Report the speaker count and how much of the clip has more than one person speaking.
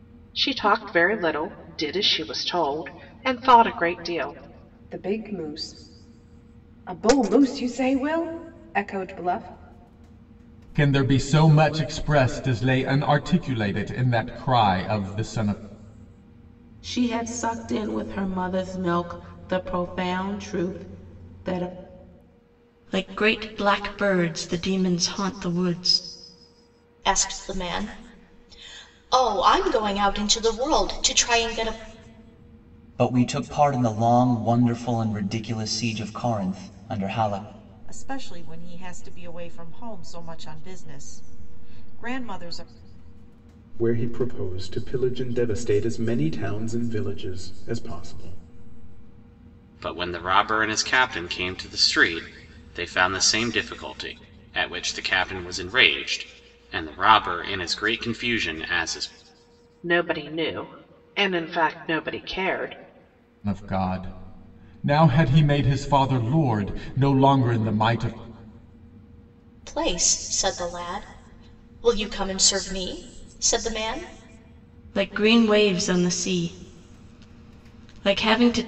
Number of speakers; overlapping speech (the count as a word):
ten, no overlap